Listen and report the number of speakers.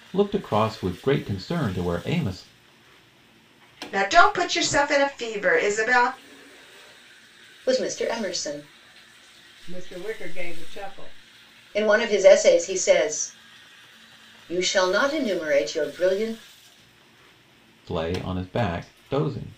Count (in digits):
4